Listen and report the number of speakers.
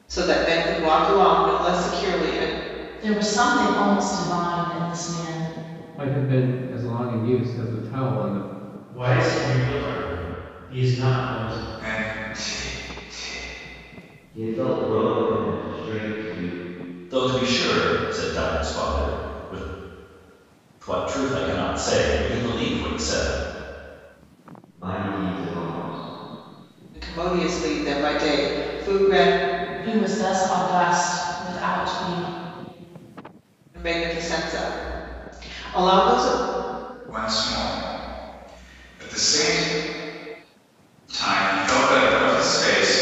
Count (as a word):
seven